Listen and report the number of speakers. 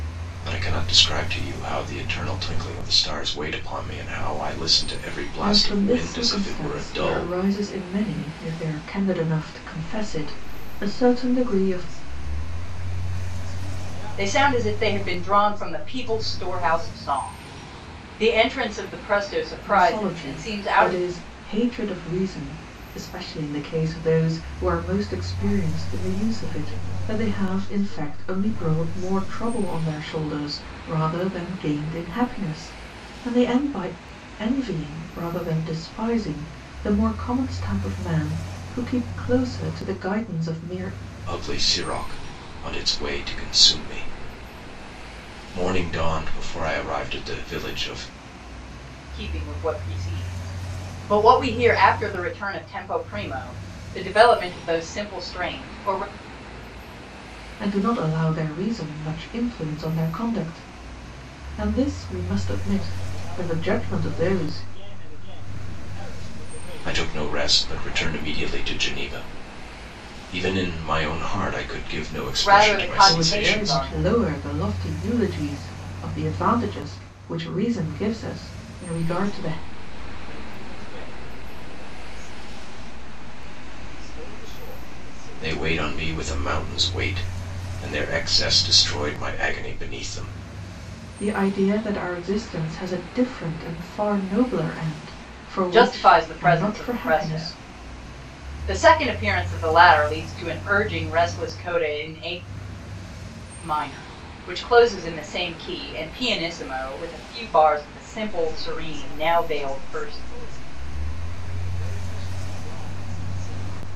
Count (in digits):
4